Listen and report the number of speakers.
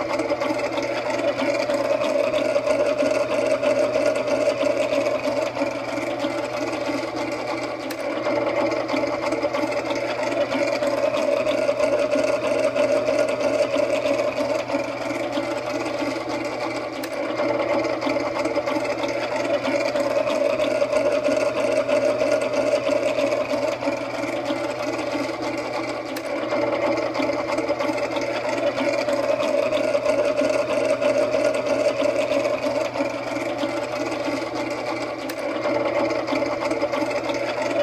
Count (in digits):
0